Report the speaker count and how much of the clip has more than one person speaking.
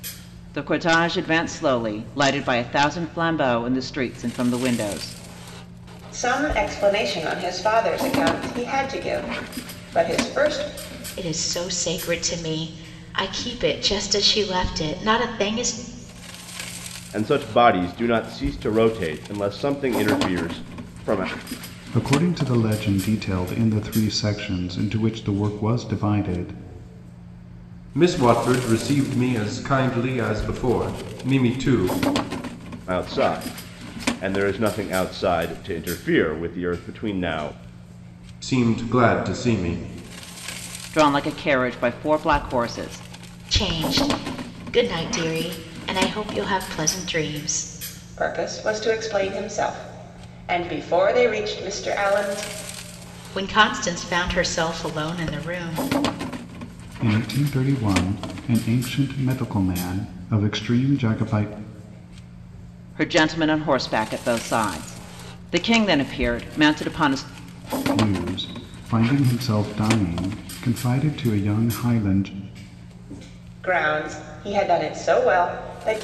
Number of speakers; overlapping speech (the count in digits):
6, no overlap